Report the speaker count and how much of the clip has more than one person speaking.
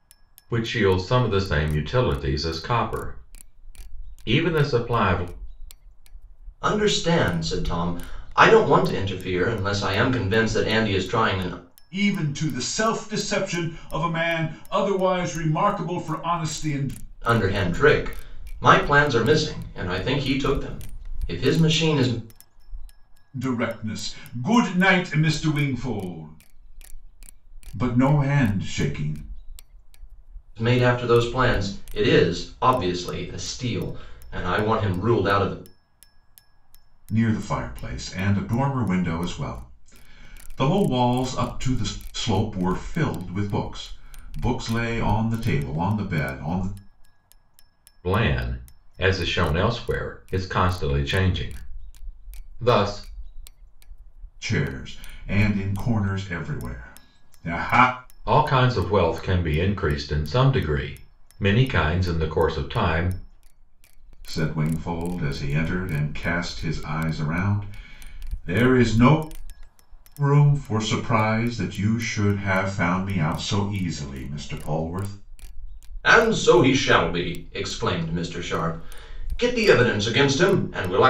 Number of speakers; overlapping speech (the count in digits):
3, no overlap